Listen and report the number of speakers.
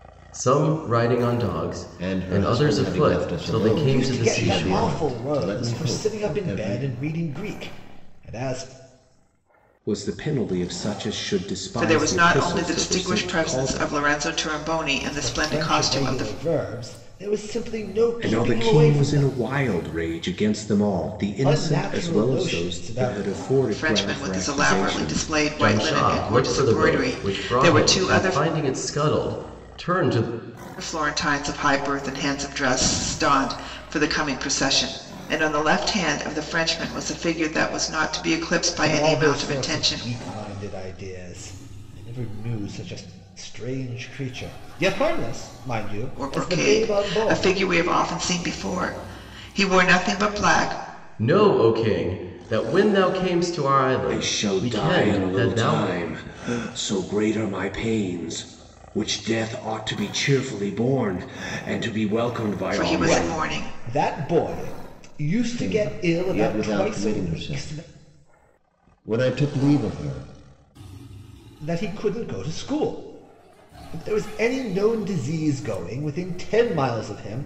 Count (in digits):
5